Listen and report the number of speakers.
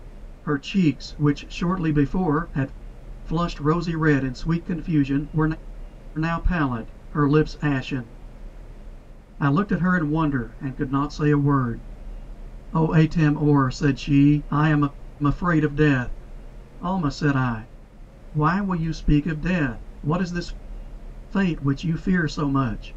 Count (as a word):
one